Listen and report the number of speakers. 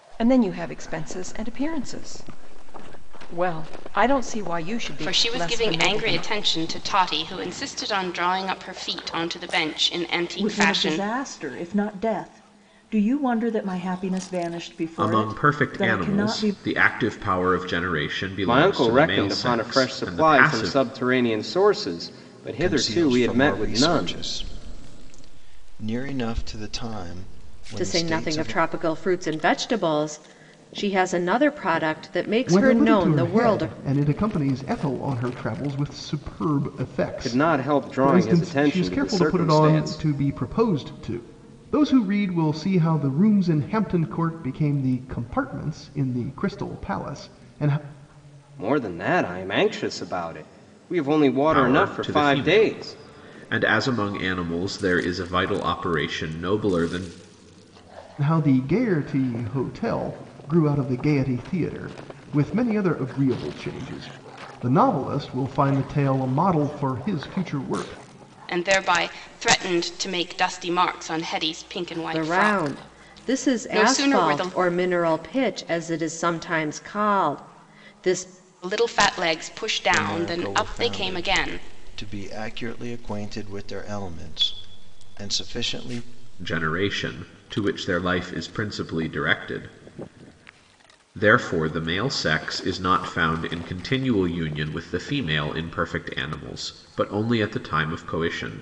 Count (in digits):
8